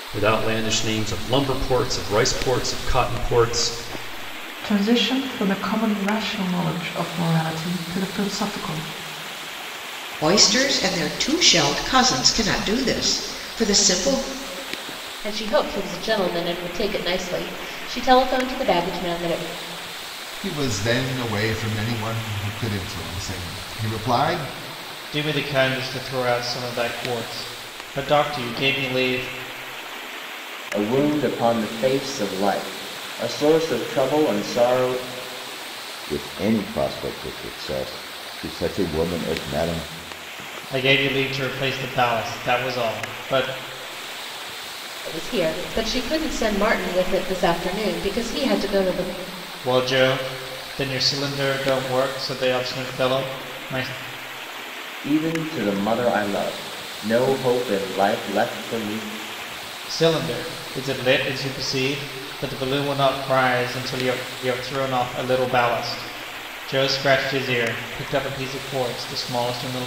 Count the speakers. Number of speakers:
8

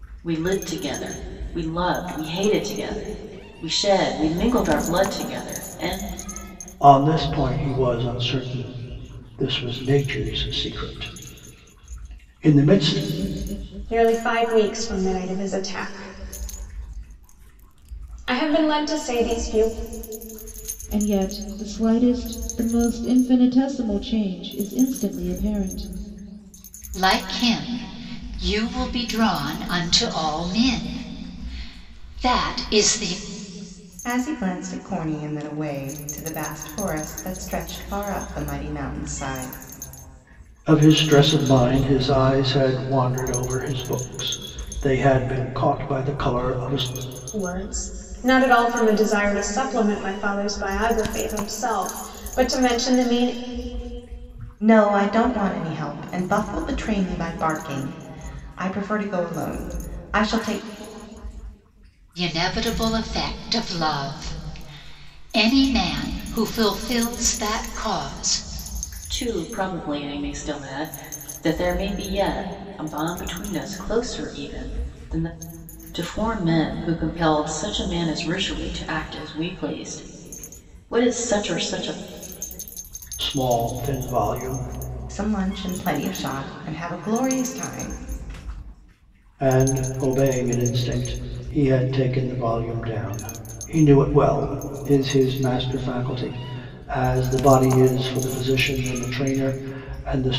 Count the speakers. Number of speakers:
6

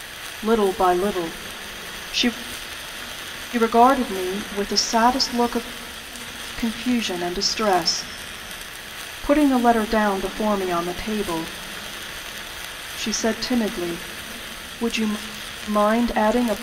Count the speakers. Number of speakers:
1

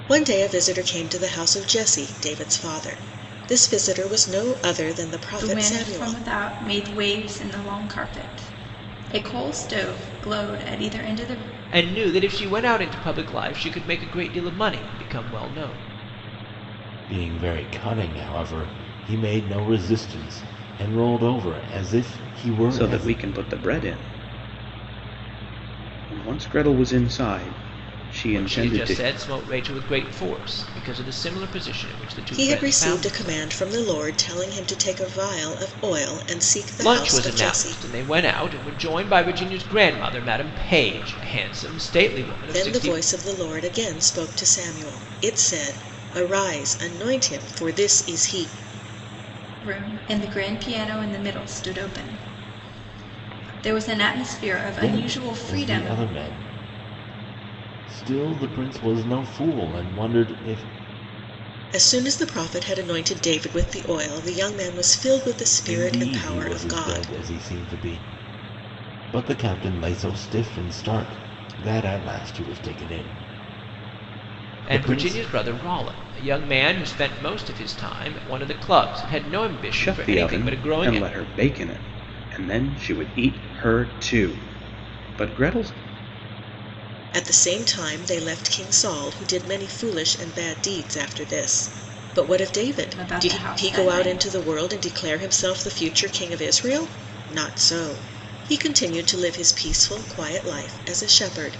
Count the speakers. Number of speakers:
5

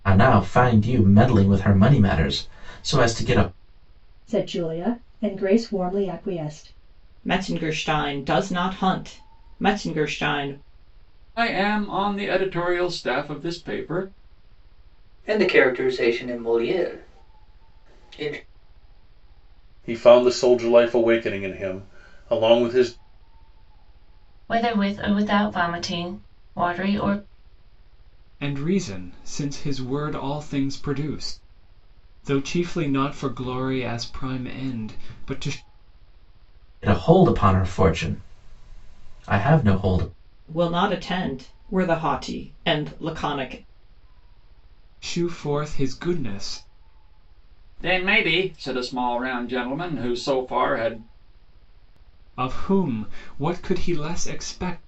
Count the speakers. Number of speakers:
8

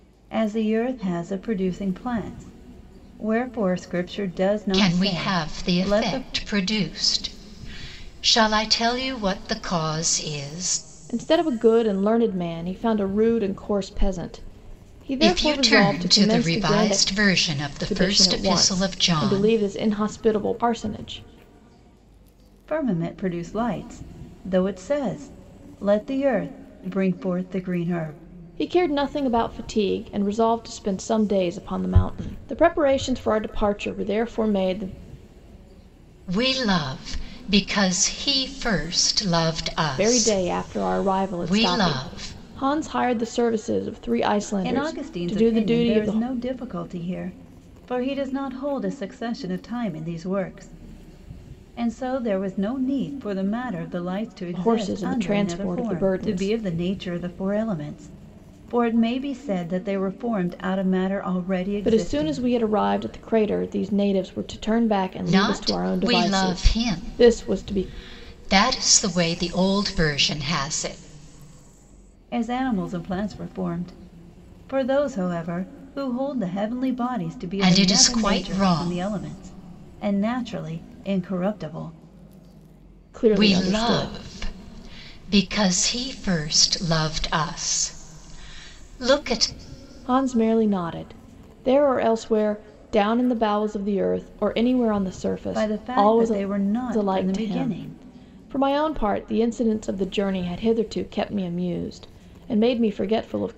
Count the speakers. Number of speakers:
3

